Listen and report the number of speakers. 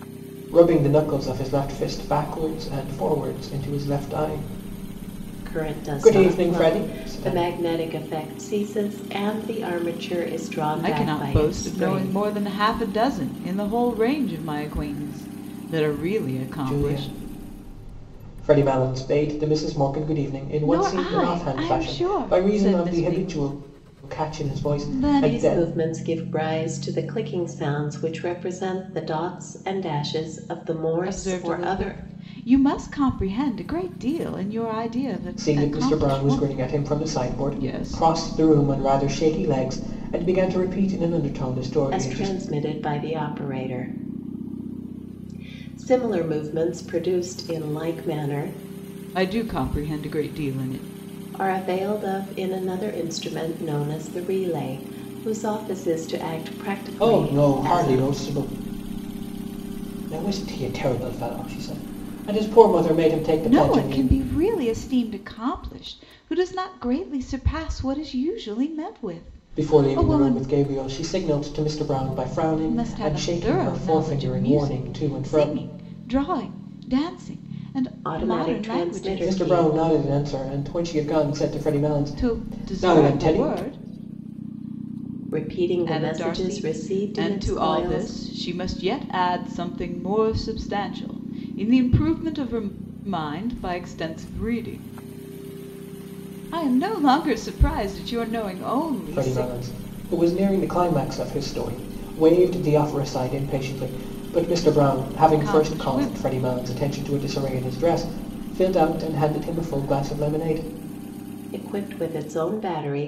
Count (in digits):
3